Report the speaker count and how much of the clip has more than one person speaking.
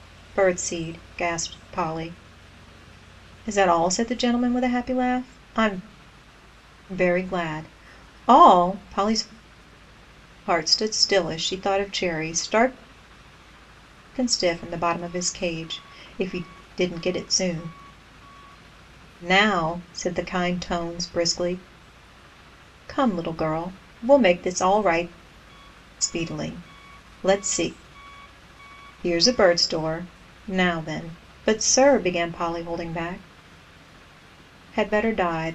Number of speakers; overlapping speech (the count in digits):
1, no overlap